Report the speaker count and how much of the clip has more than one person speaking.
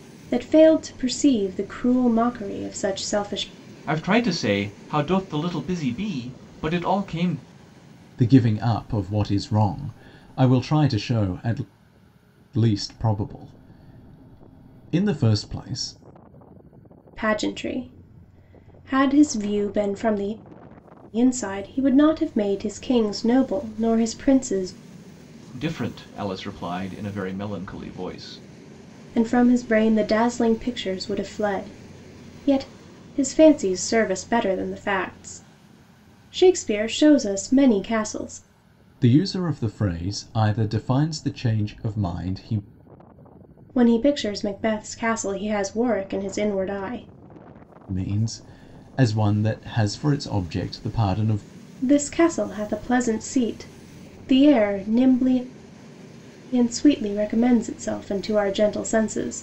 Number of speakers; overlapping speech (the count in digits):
3, no overlap